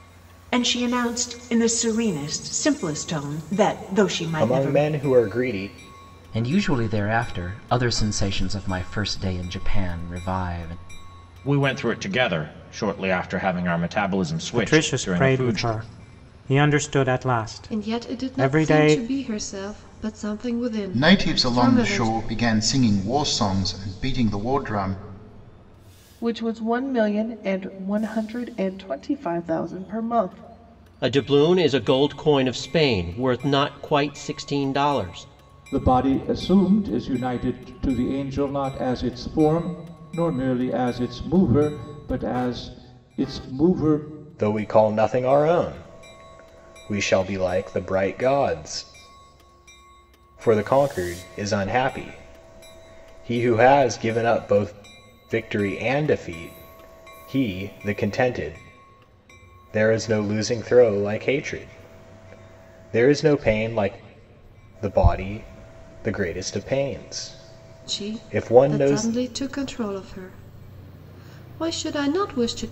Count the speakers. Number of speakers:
10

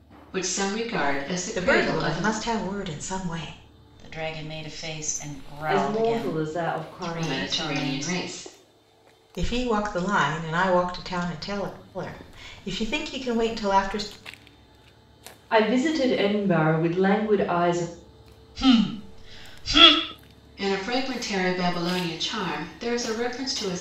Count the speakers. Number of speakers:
4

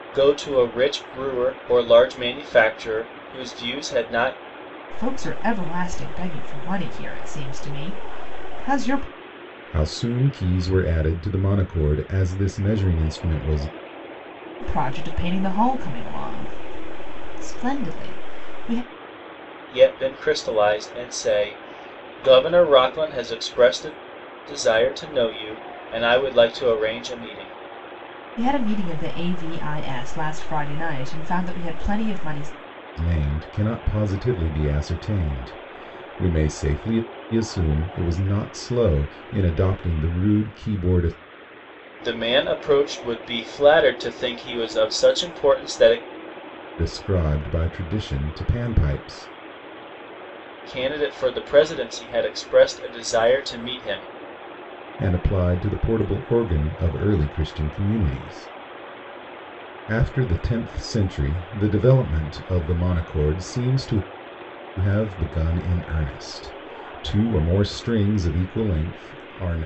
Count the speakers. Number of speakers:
3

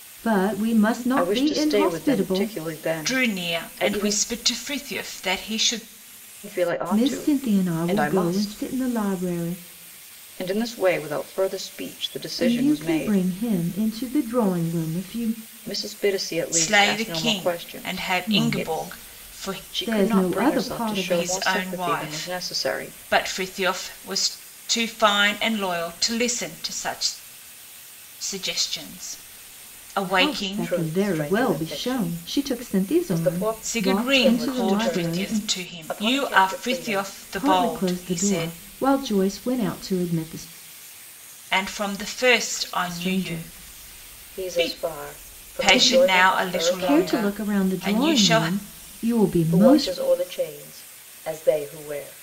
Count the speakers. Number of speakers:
3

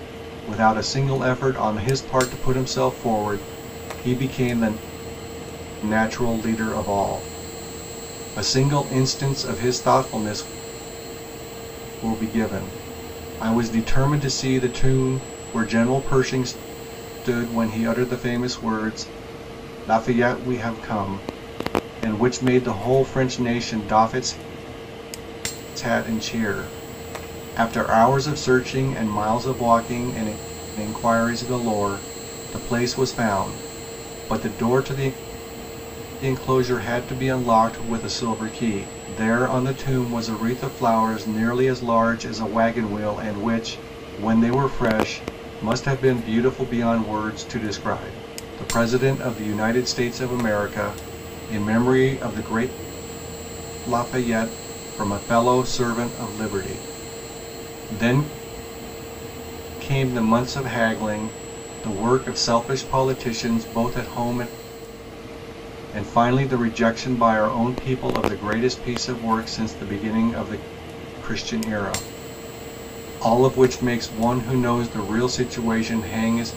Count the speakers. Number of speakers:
1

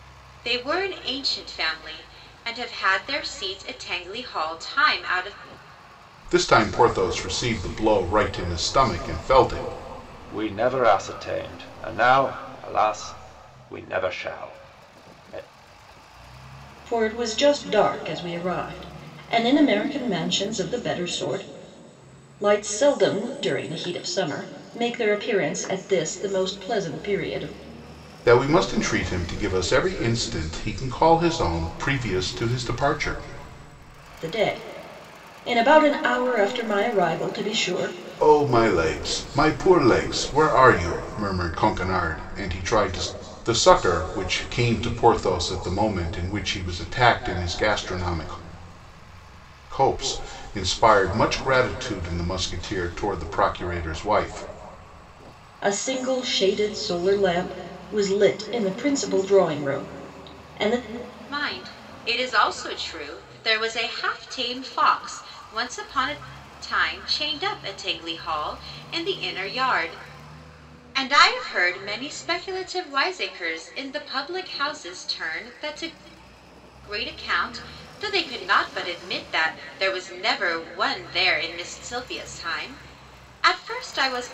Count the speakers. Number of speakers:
4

